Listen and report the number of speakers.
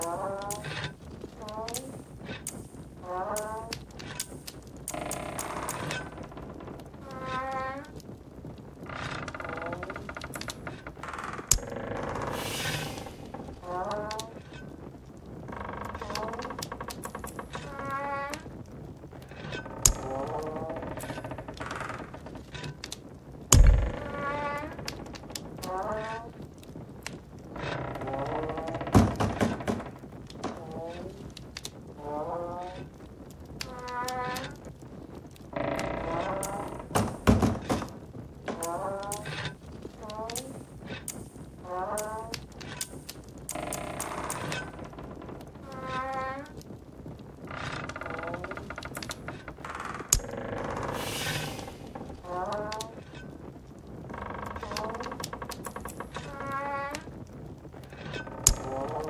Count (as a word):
zero